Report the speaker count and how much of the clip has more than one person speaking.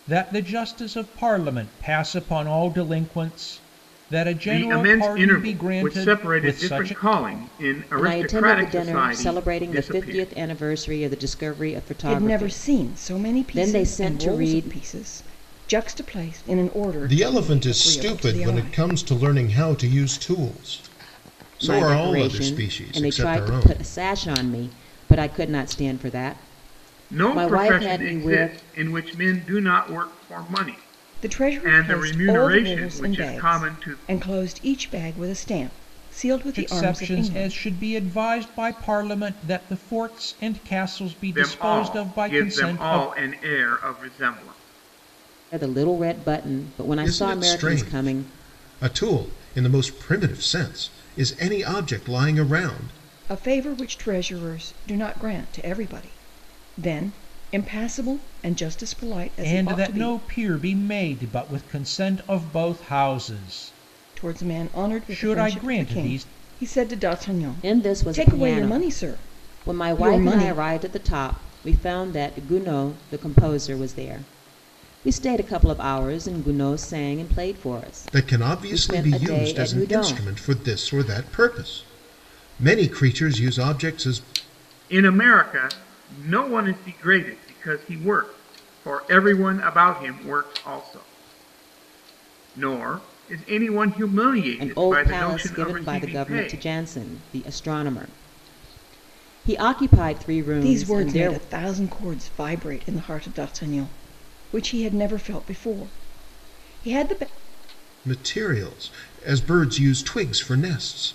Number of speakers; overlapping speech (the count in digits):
5, about 28%